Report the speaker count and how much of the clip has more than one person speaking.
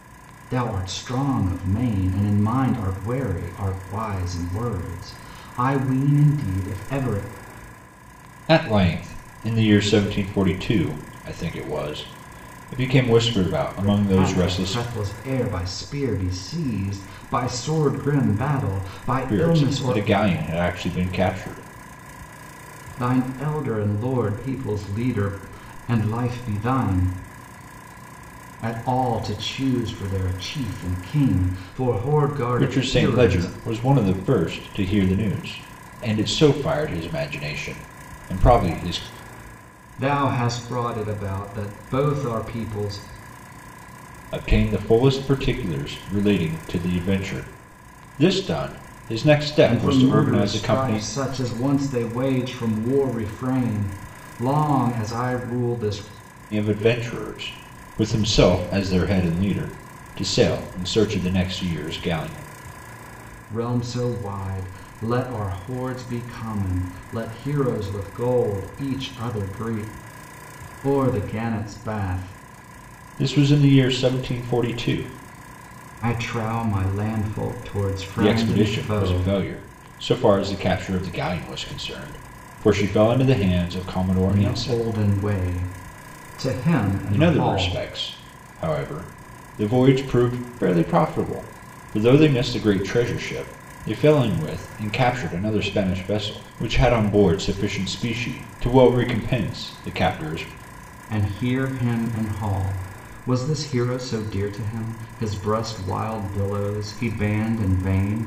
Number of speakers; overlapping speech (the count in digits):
2, about 6%